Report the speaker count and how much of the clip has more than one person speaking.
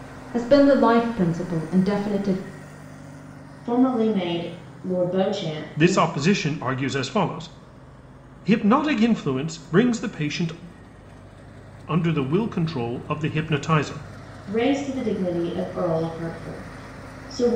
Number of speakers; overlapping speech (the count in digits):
3, about 2%